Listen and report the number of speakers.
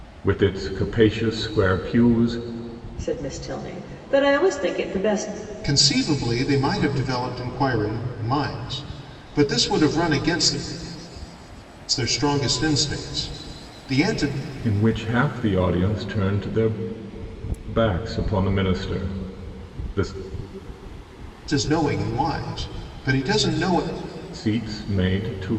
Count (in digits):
3